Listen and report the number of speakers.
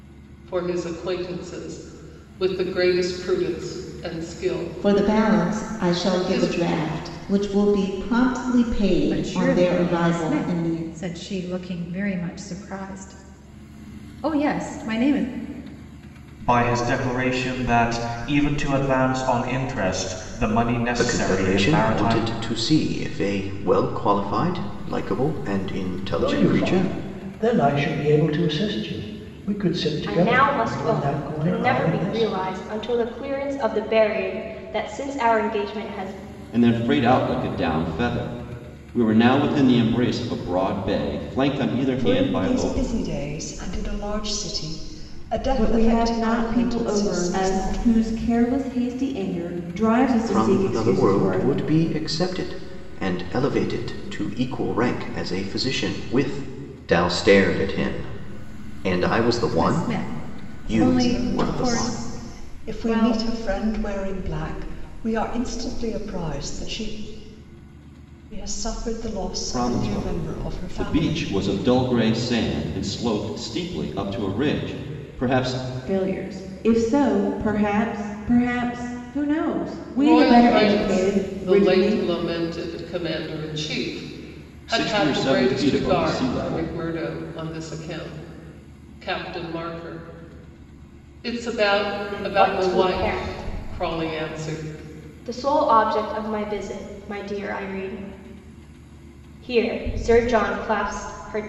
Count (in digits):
10